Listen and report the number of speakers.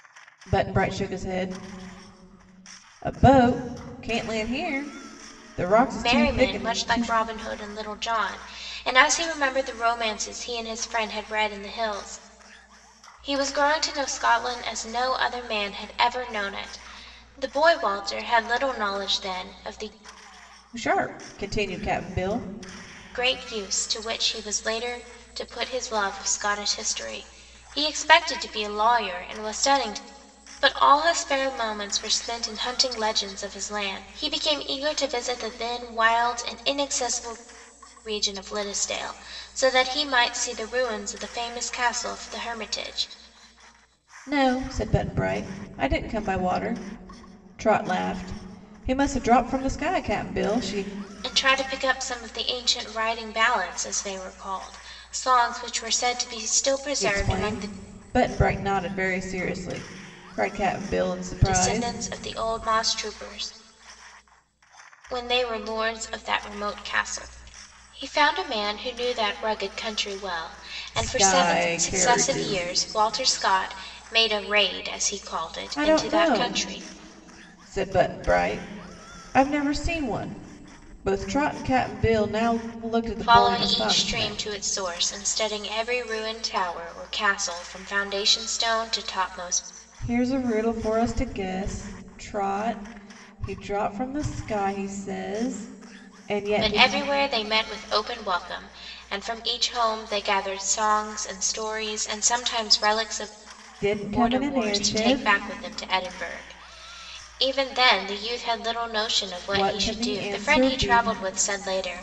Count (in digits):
2